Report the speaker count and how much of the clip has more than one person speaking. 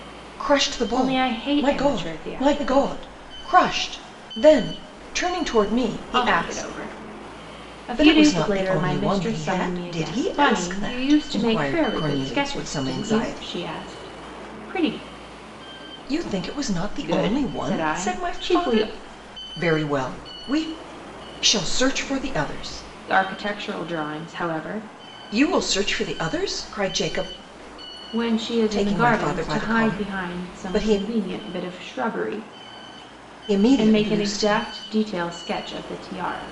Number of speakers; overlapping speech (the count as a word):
two, about 37%